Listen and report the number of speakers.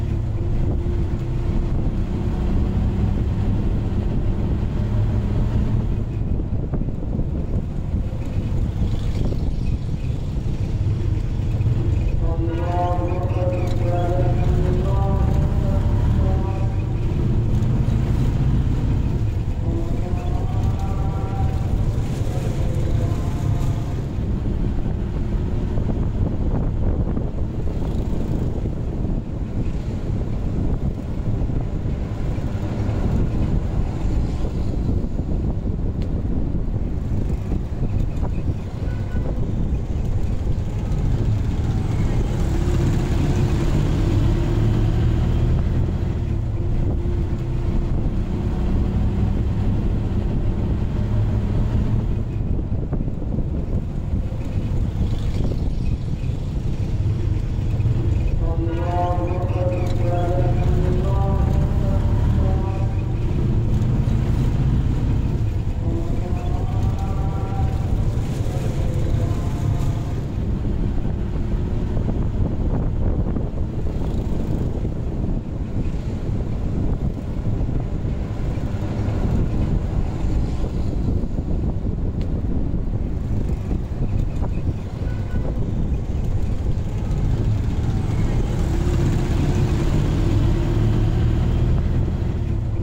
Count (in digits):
0